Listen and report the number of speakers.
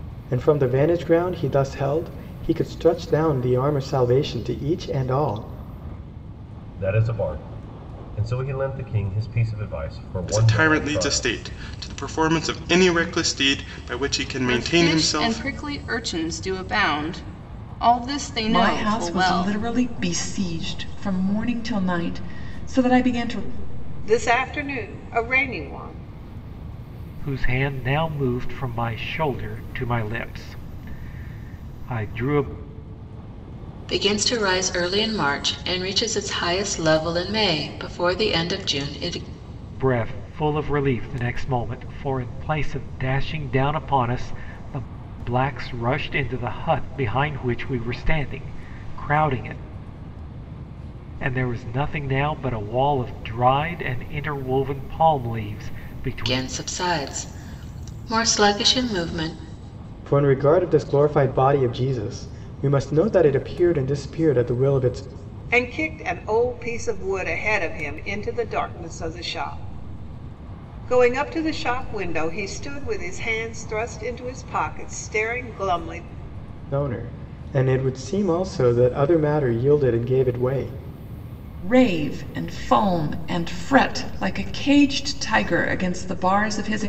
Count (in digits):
8